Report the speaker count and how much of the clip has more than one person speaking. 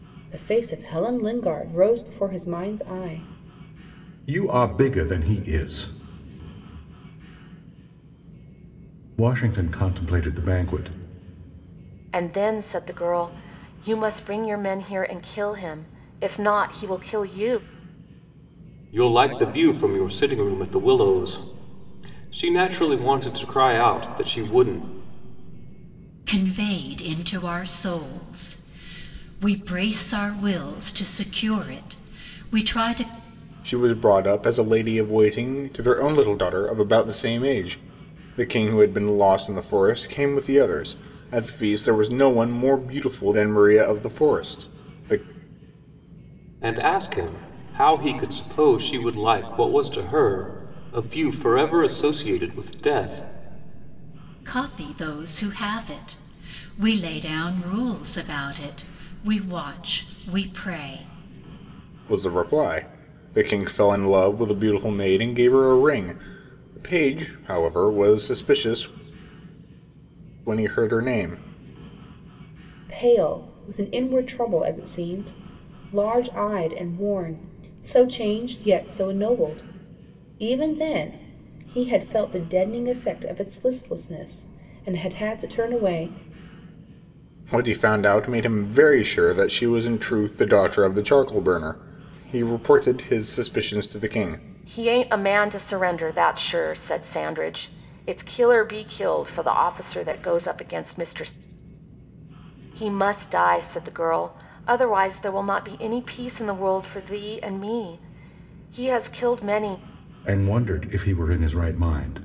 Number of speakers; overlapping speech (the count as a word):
six, no overlap